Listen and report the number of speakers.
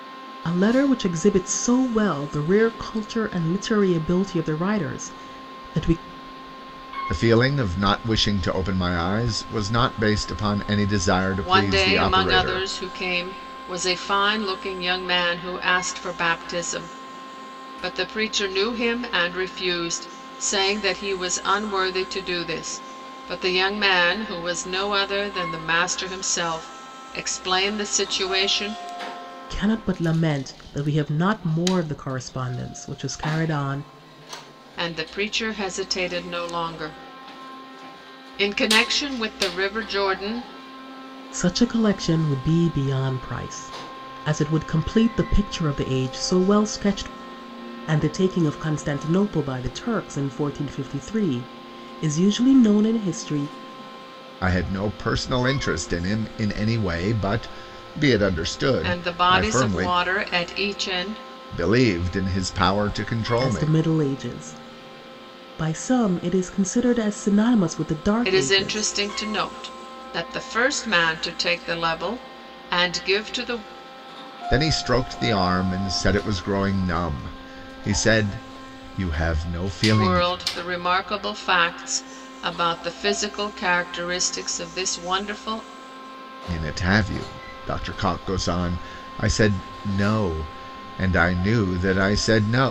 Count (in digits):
3